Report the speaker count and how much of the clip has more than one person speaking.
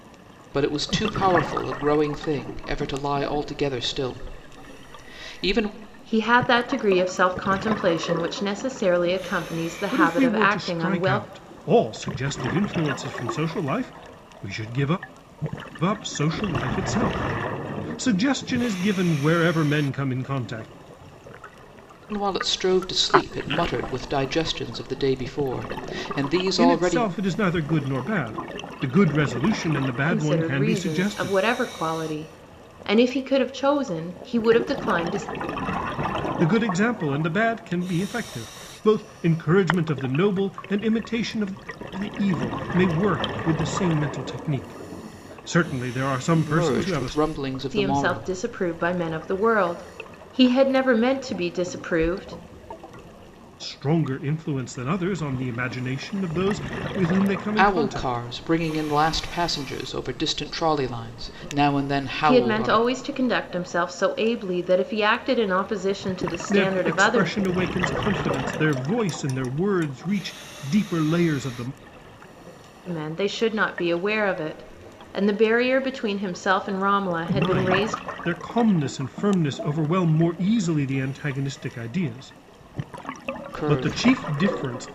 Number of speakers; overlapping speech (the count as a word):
three, about 10%